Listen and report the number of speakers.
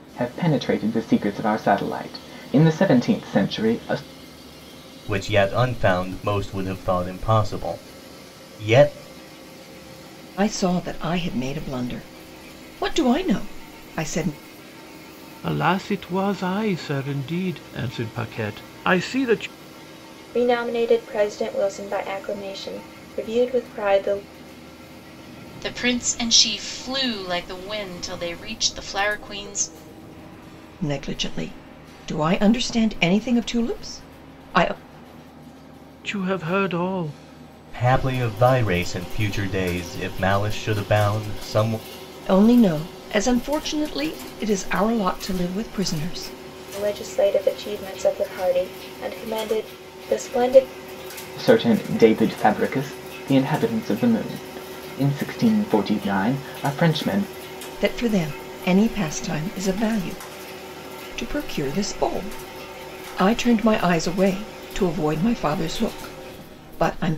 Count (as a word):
six